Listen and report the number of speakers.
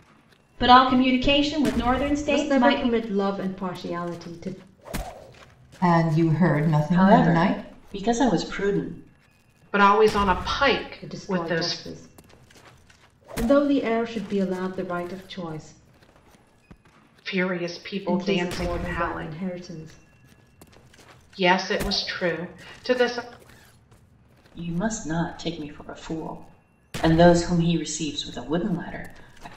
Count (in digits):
5